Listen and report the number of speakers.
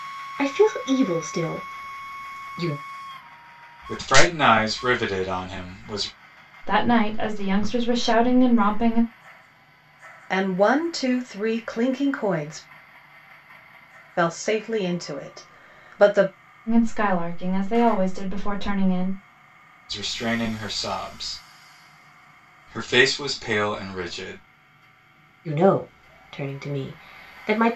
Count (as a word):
four